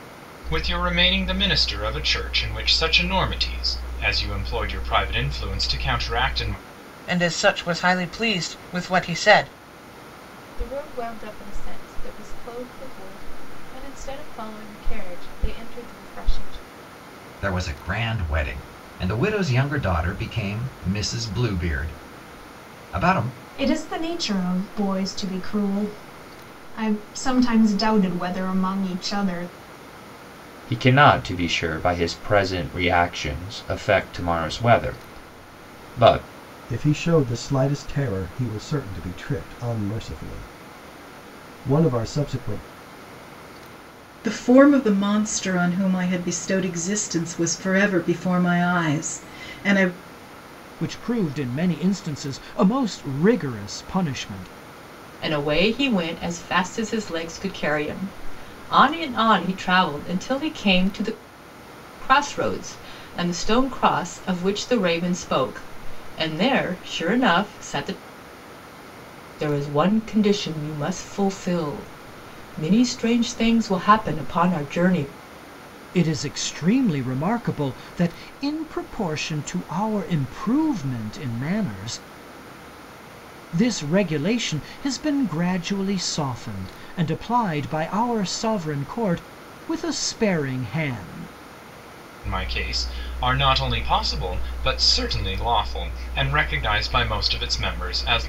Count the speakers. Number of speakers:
ten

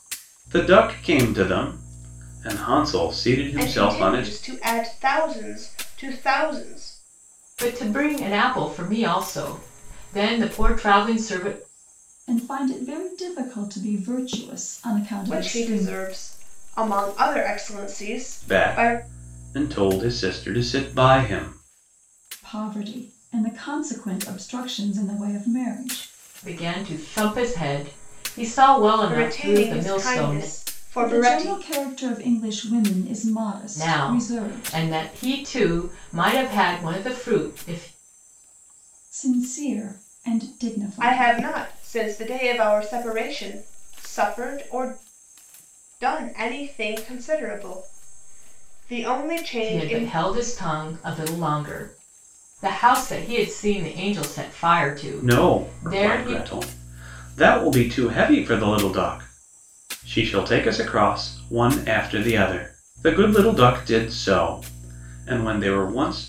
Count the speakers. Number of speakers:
four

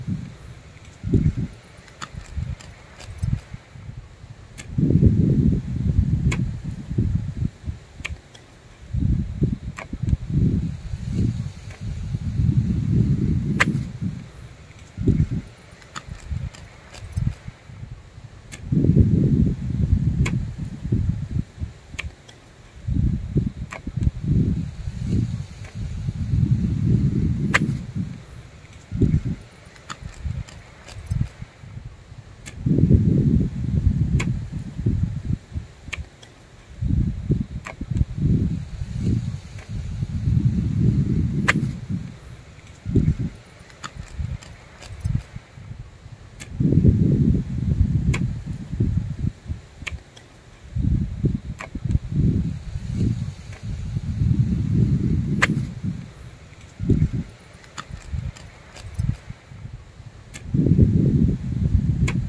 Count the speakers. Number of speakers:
zero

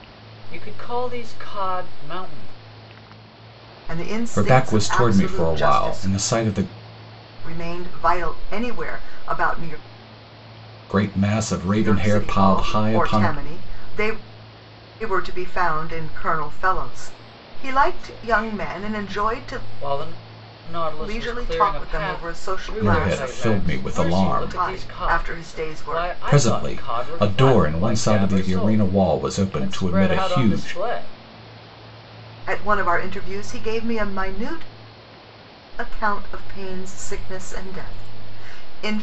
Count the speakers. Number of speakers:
three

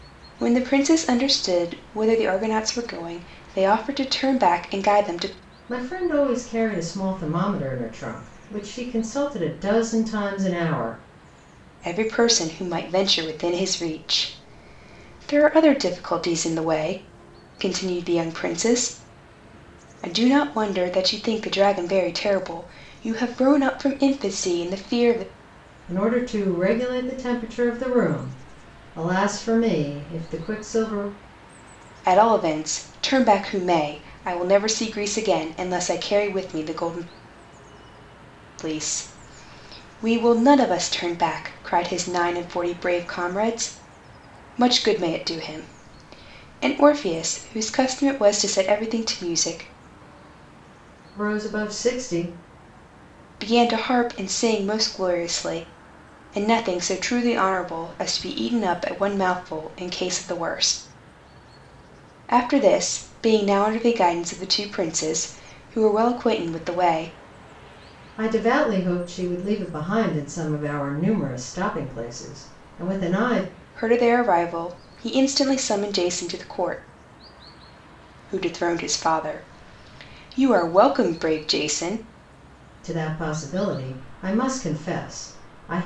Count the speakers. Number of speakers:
two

